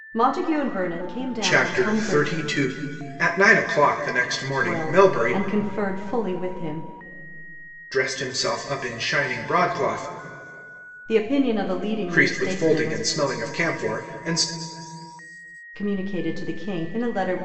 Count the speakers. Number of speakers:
two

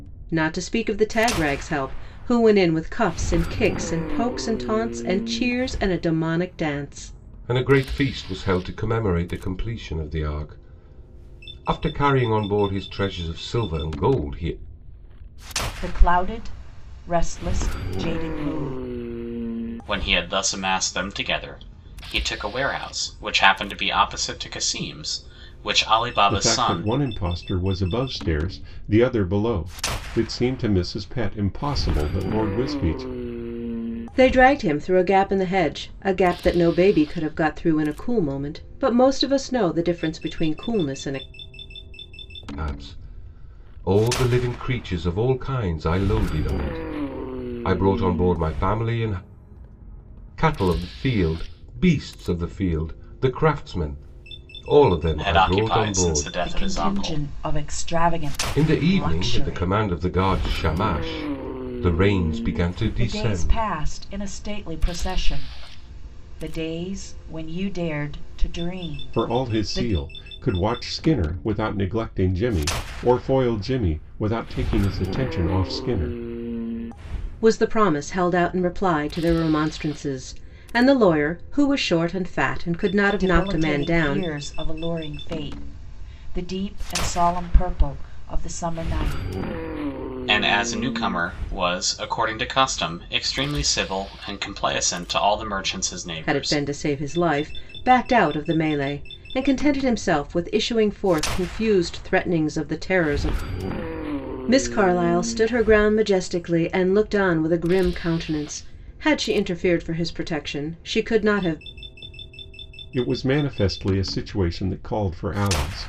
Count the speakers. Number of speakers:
five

